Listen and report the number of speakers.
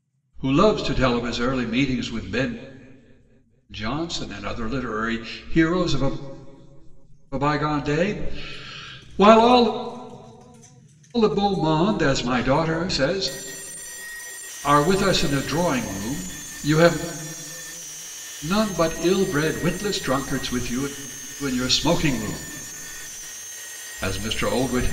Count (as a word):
one